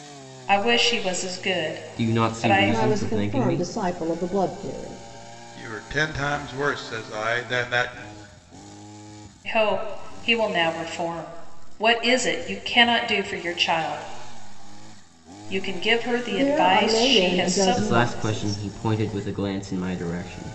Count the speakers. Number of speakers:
four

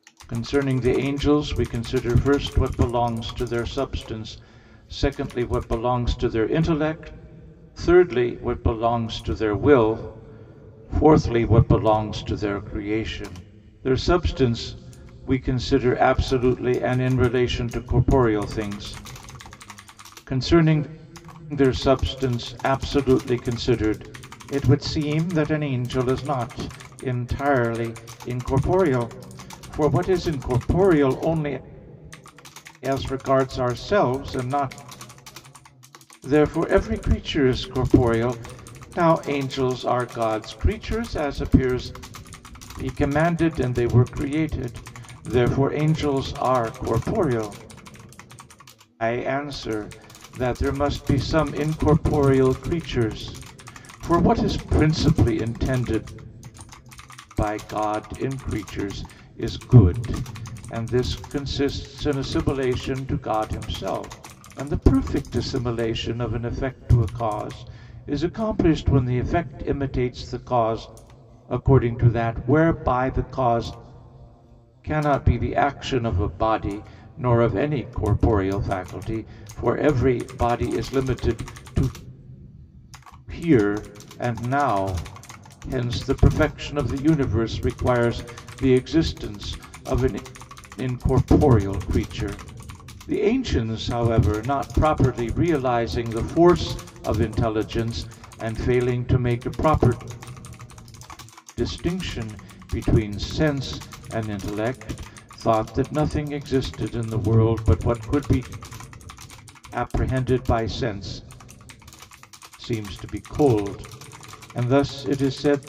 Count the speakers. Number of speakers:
one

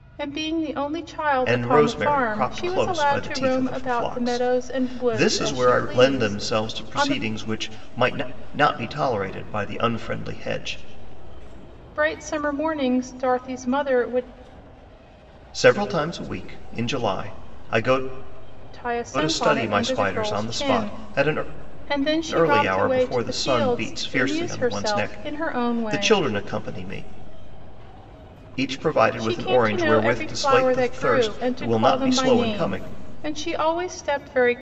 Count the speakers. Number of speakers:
two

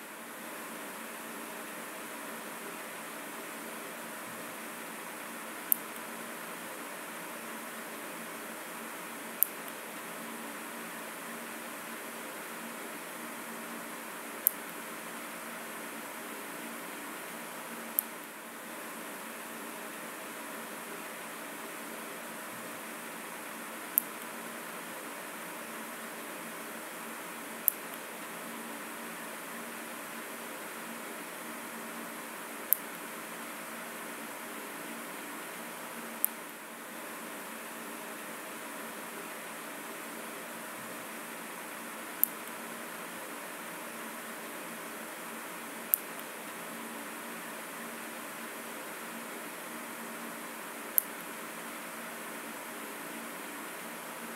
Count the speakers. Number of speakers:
zero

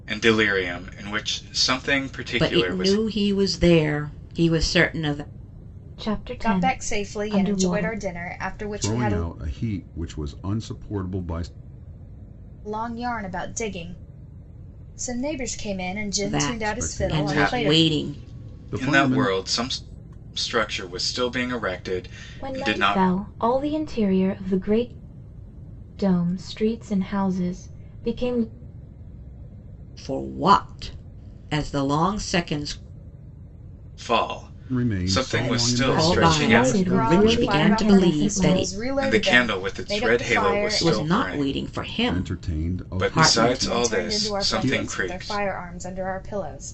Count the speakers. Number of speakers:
five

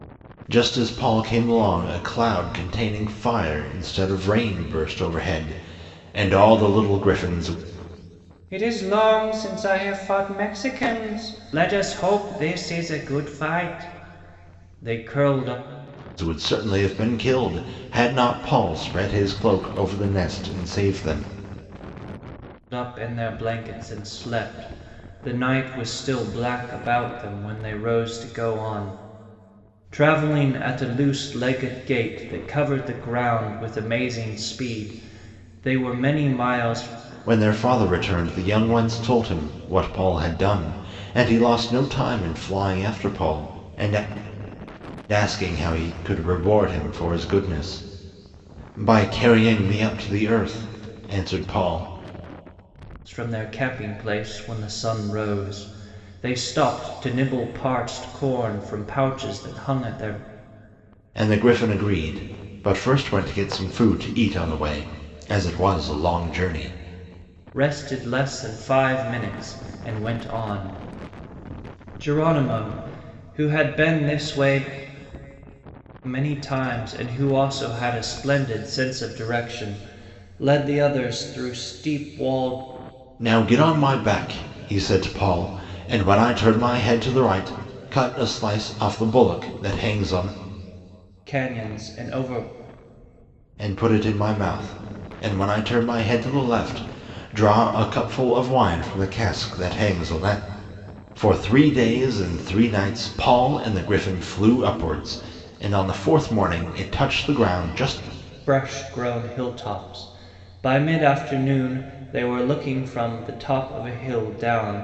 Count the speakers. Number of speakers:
two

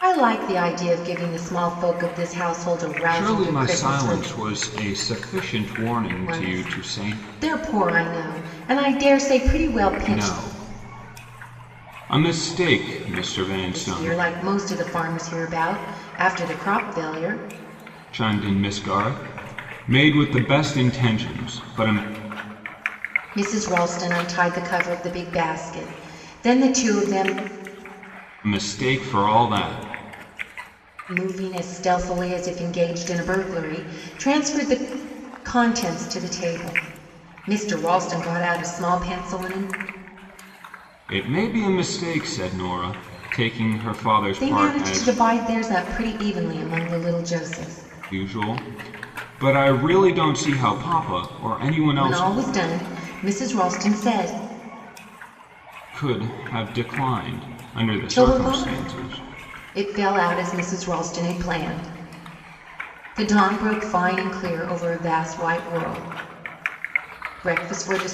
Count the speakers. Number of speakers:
two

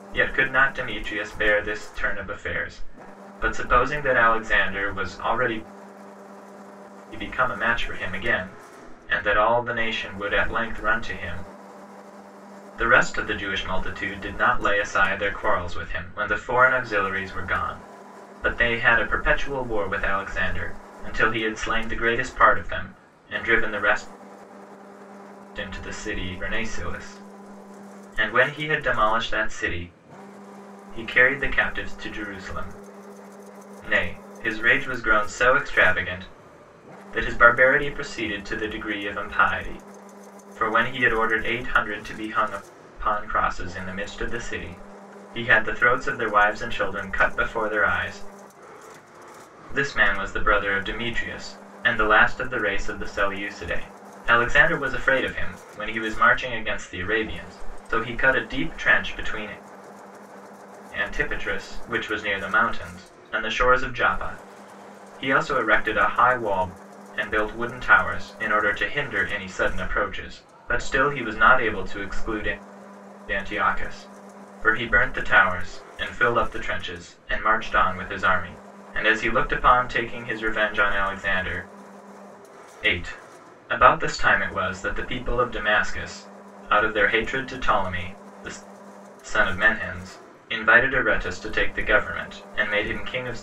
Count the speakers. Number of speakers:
one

